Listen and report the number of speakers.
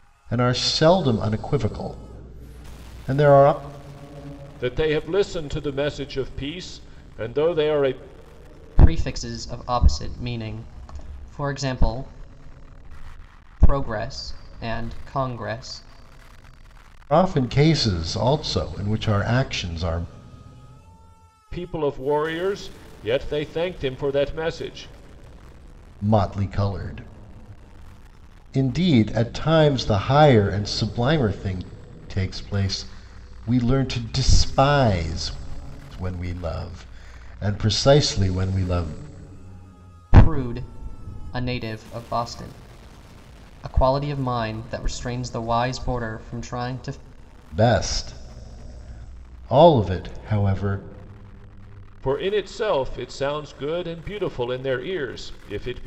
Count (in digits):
3